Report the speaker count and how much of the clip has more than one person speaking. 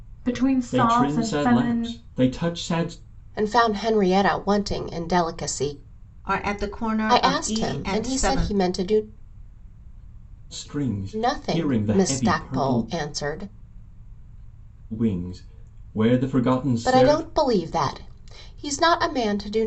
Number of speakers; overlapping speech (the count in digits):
4, about 26%